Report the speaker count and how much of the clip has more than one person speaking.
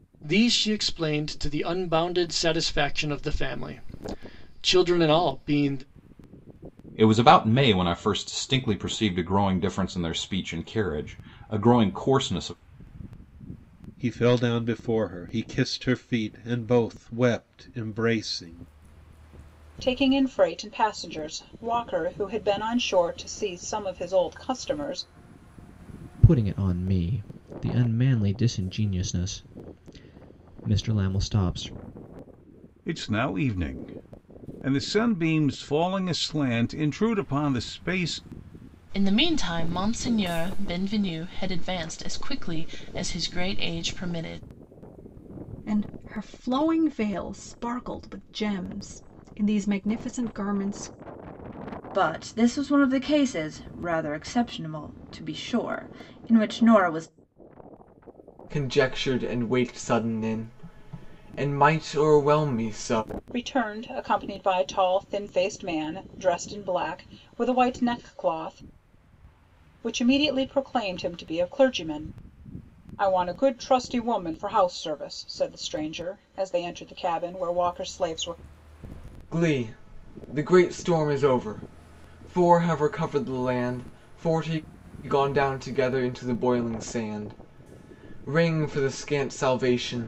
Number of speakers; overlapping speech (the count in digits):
10, no overlap